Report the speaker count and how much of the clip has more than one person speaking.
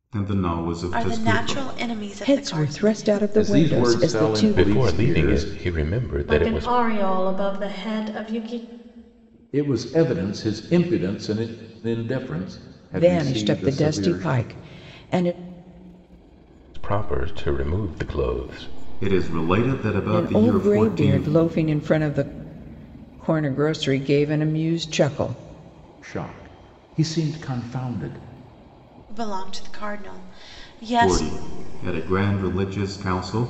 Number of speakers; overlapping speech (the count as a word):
six, about 22%